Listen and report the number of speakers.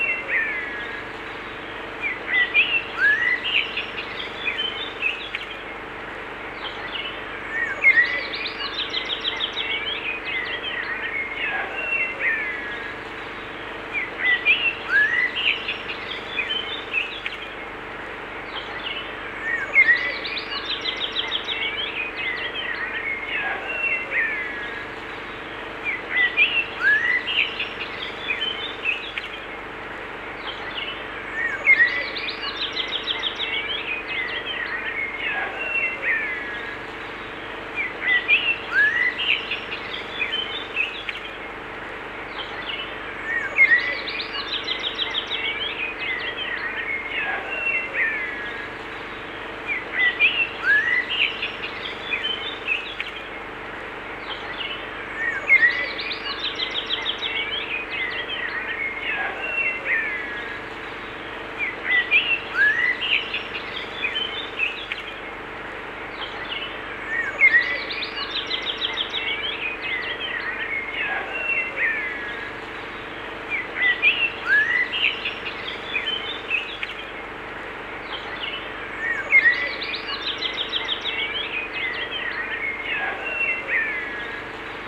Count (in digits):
0